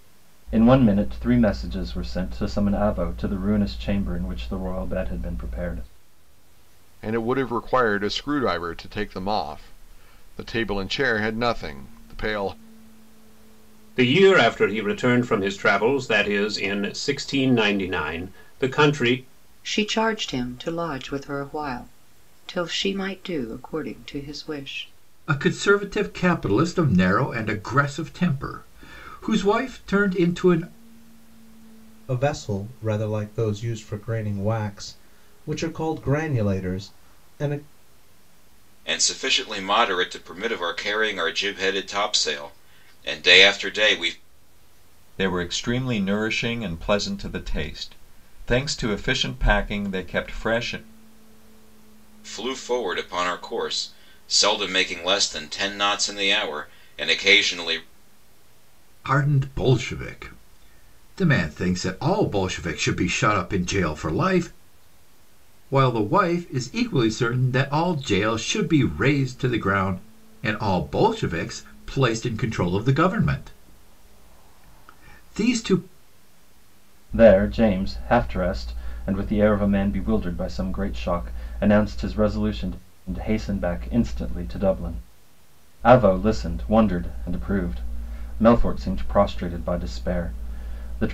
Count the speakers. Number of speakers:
eight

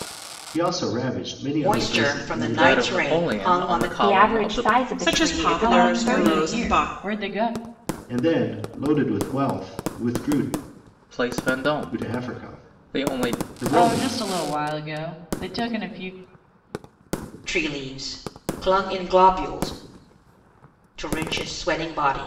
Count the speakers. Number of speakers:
six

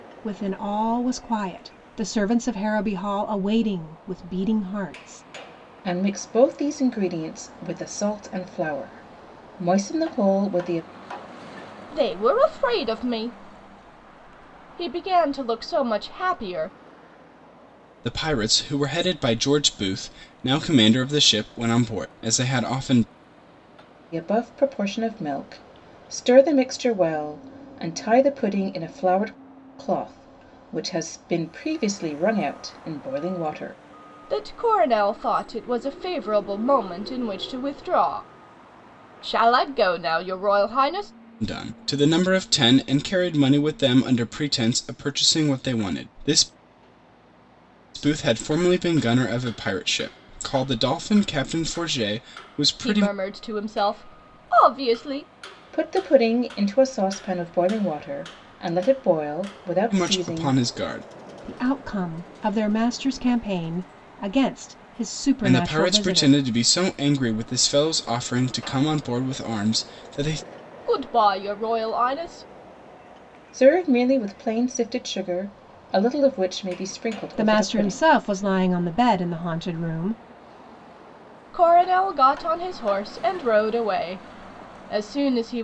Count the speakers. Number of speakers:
four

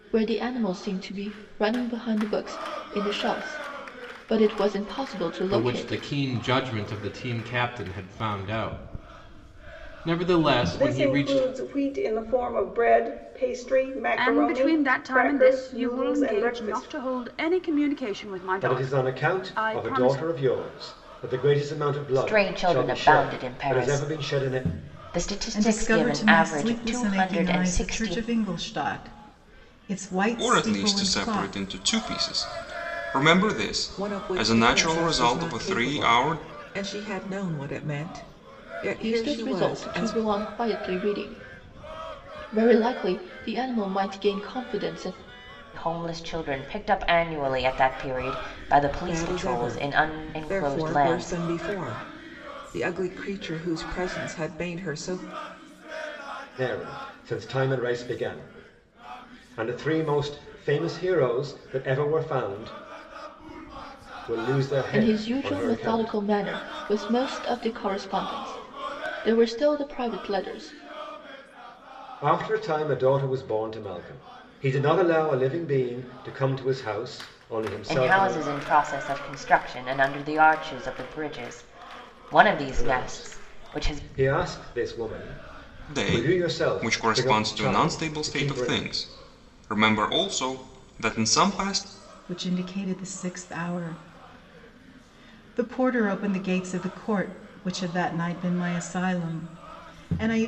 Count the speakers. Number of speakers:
nine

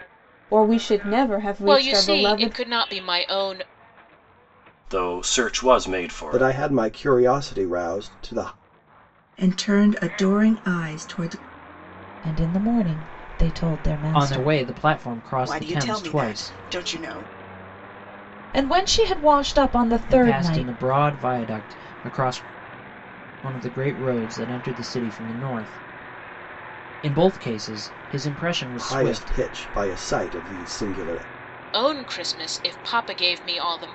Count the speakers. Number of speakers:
eight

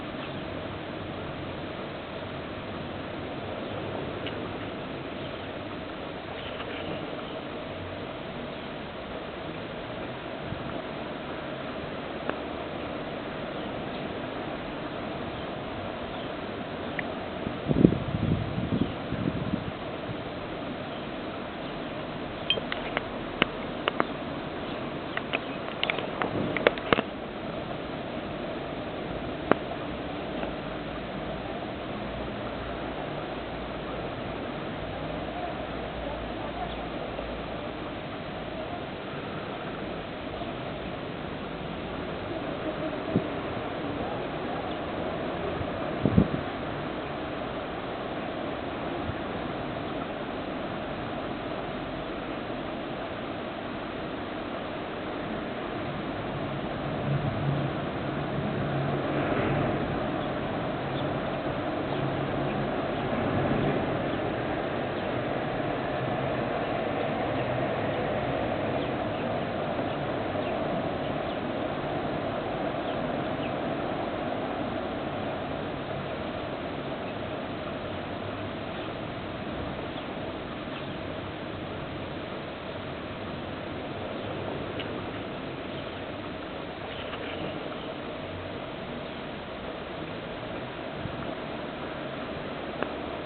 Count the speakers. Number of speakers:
zero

